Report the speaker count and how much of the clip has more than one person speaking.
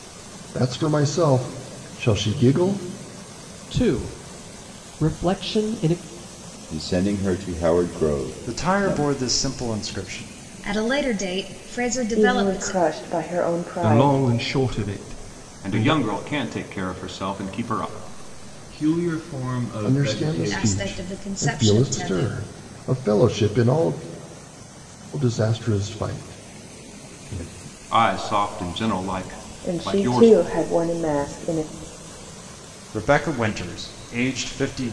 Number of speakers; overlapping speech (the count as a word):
nine, about 16%